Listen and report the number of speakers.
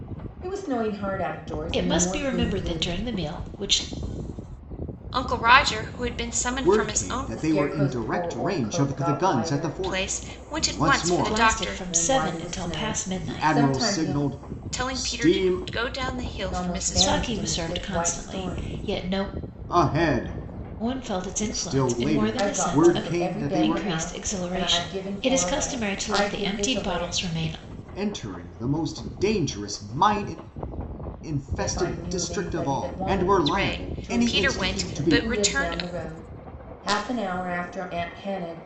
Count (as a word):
four